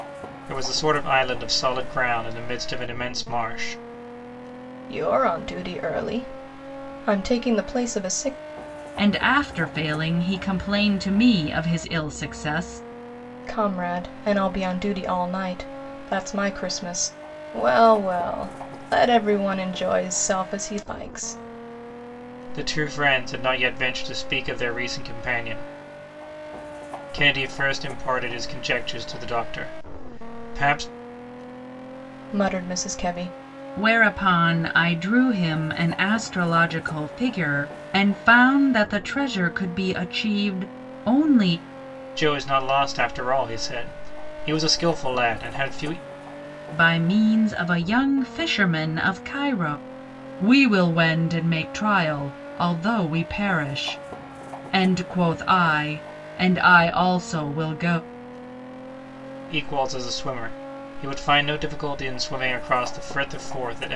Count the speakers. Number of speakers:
three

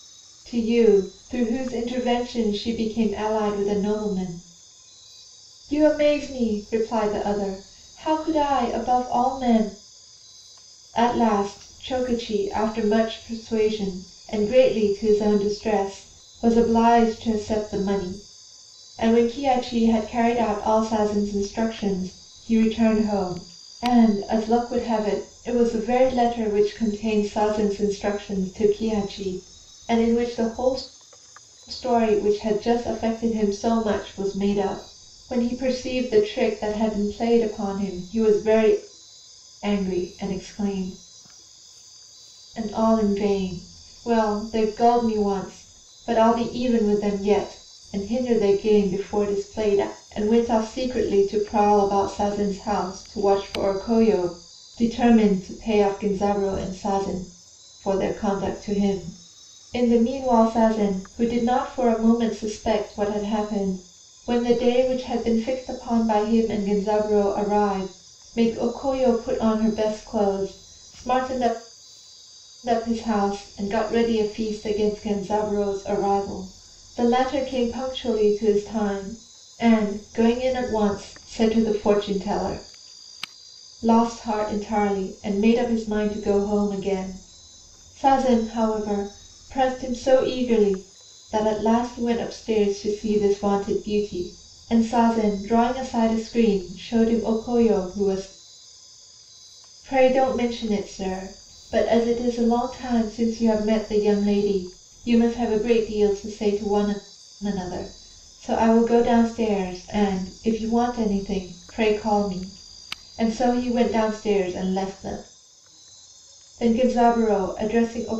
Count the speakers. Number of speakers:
one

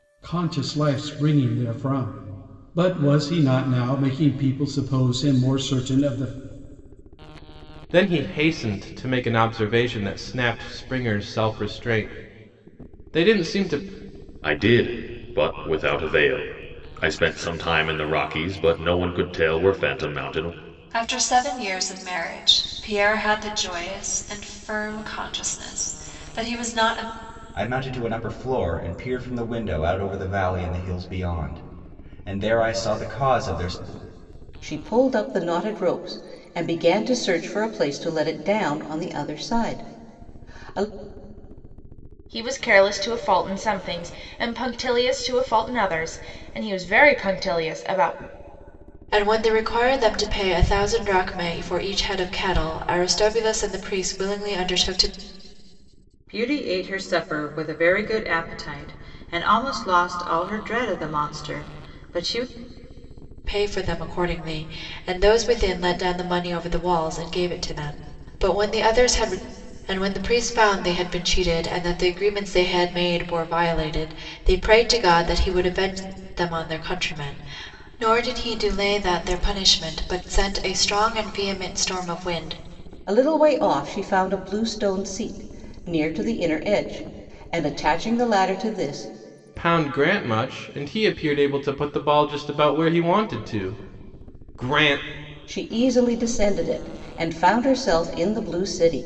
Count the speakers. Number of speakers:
nine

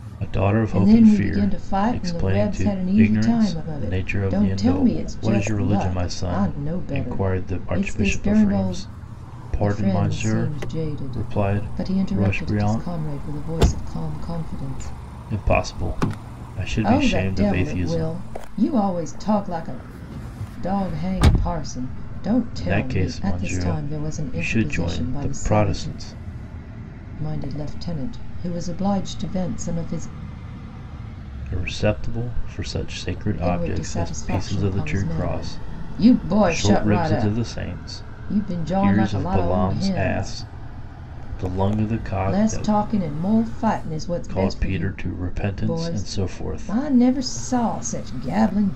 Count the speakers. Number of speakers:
two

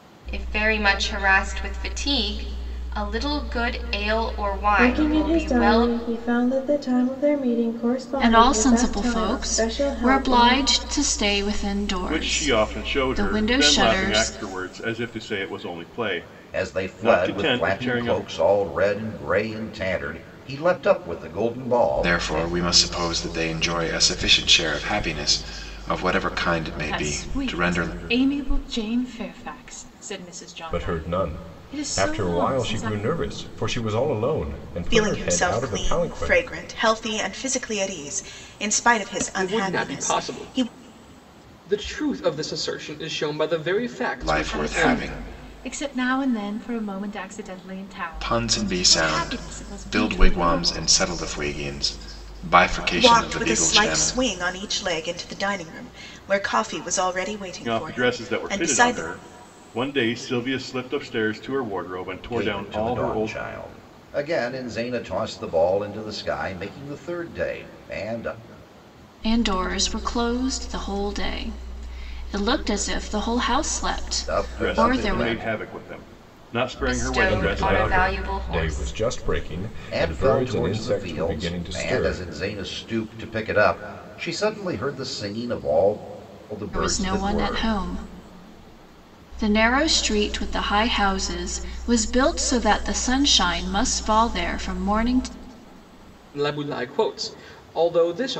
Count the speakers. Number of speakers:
ten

